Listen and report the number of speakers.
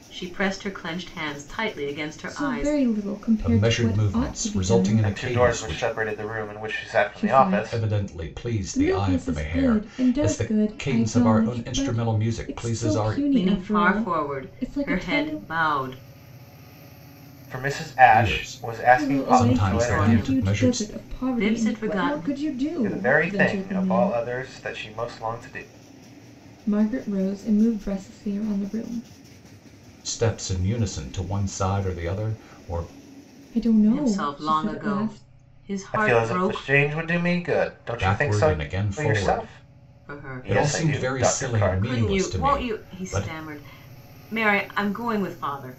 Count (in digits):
4